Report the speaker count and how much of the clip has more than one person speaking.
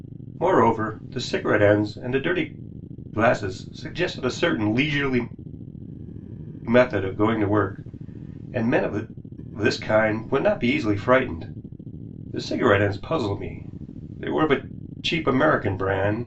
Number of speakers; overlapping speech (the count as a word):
one, no overlap